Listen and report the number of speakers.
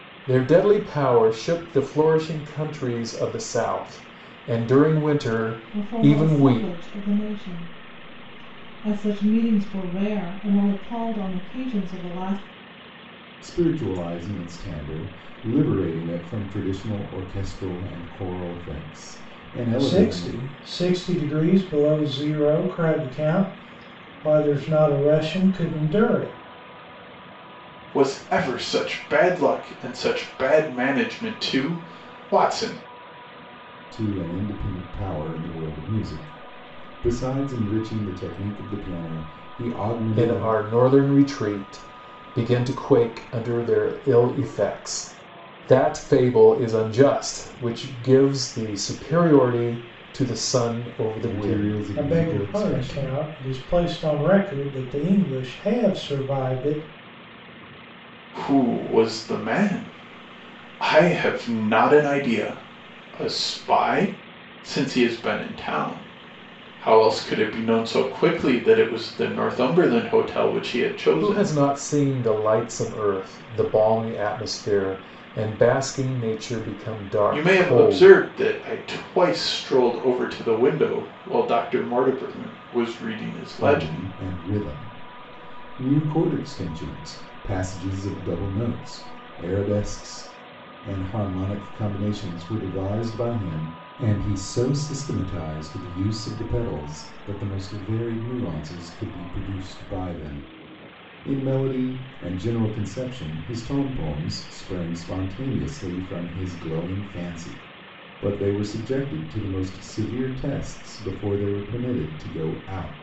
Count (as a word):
five